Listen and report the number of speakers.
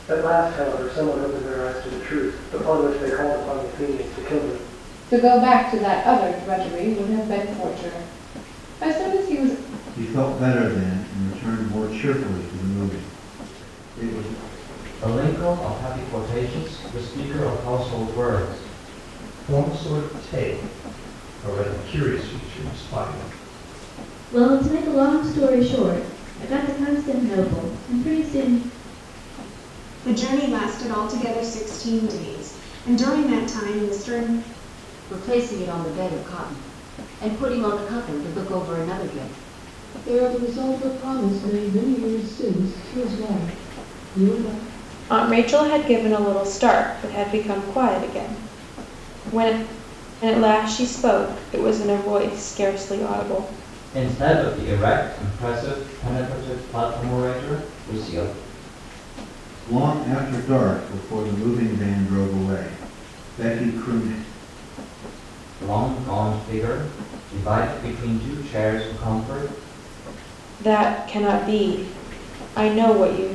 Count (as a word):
ten